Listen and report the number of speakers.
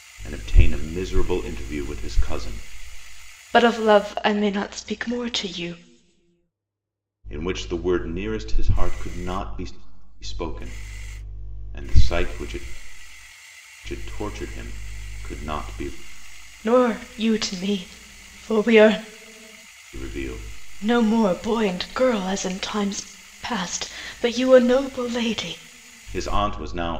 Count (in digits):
2